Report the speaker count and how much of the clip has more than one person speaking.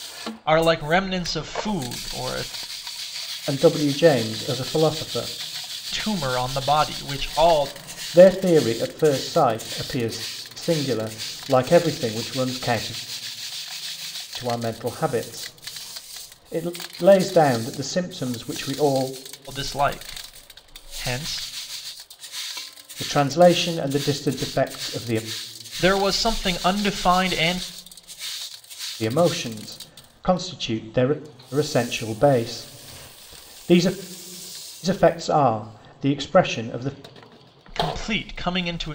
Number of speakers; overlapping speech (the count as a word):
two, no overlap